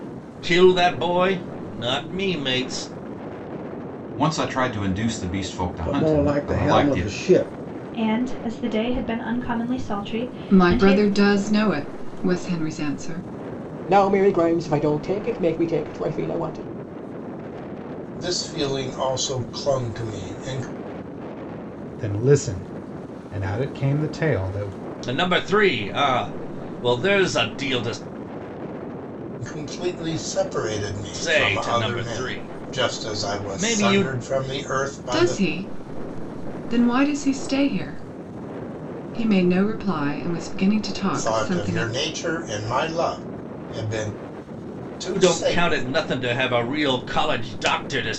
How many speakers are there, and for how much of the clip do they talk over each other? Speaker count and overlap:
8, about 13%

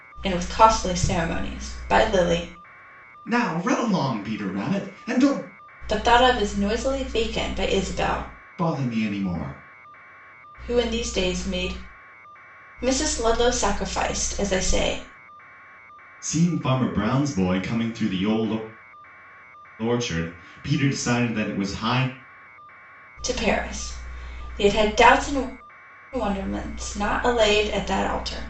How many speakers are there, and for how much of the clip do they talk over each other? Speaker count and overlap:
2, no overlap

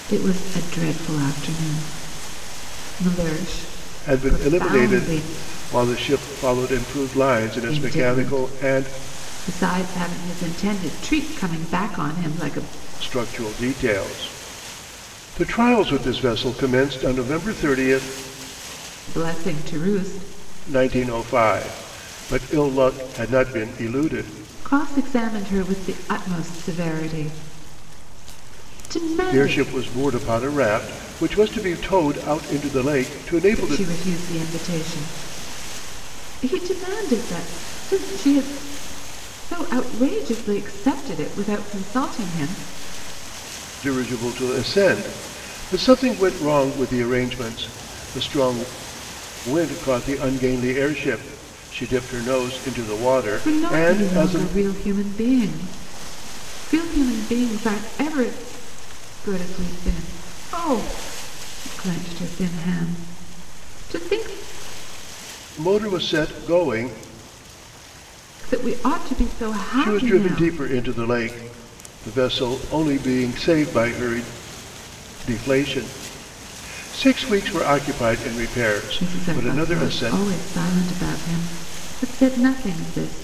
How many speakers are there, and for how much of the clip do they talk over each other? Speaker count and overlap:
2, about 8%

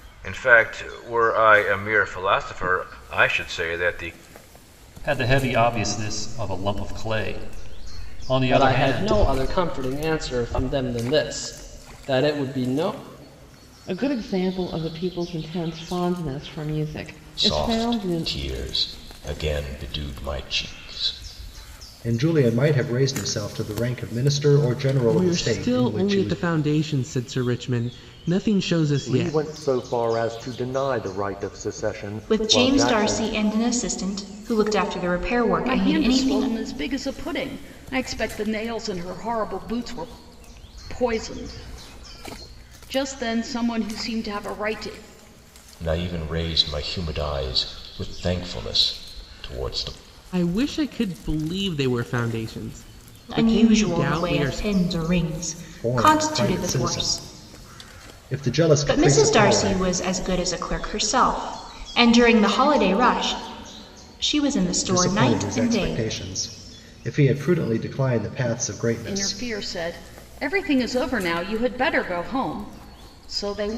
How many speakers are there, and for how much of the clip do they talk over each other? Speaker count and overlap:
10, about 15%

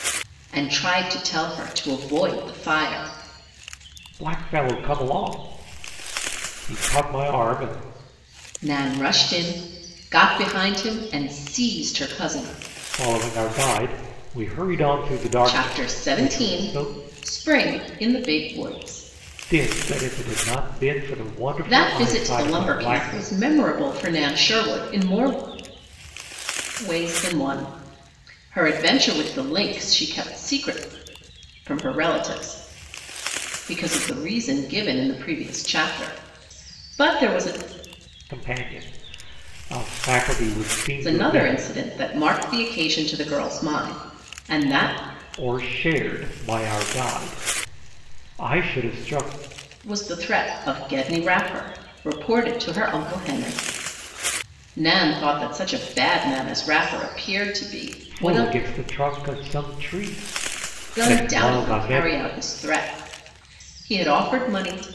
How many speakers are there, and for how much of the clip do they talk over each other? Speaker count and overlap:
2, about 8%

